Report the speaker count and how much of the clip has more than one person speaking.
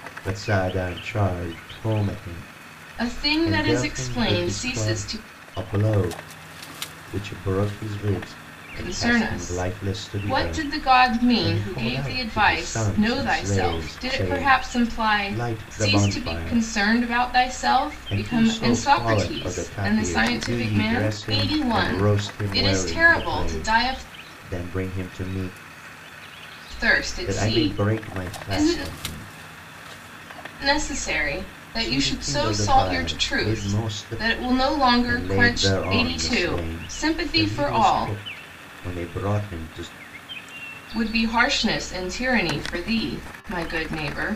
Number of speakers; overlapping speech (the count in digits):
2, about 50%